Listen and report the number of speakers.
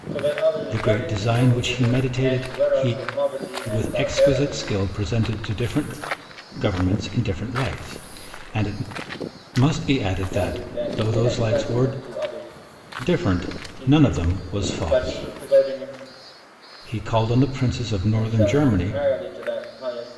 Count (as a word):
two